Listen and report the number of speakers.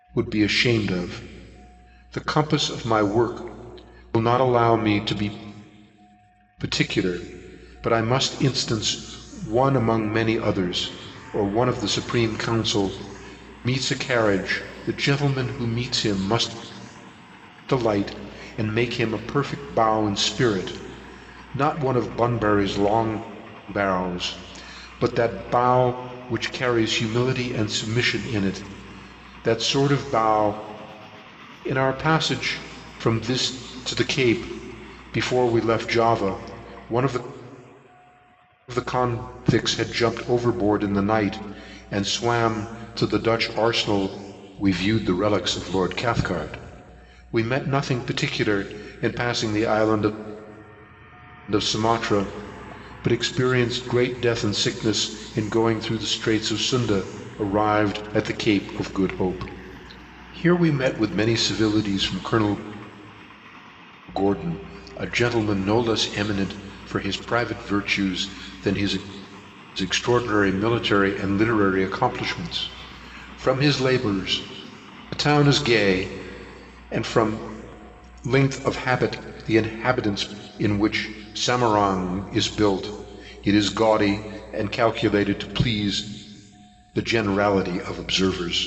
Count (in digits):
1